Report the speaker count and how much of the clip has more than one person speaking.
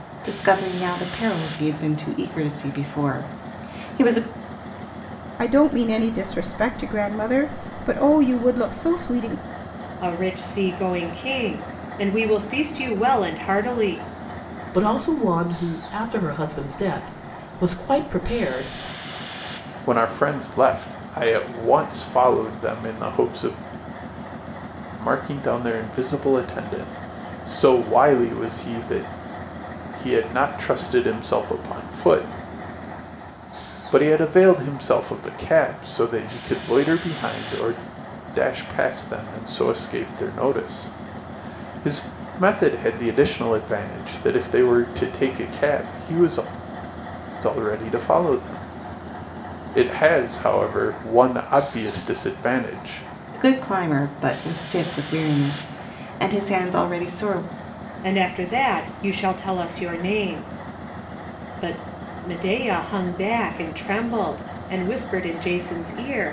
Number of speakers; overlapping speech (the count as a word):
five, no overlap